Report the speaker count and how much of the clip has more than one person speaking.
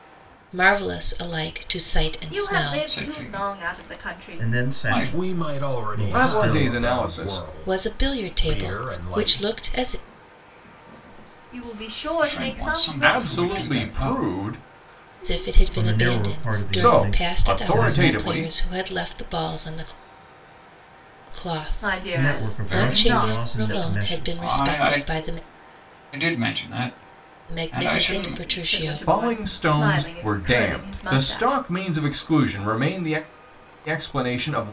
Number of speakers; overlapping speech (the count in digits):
6, about 56%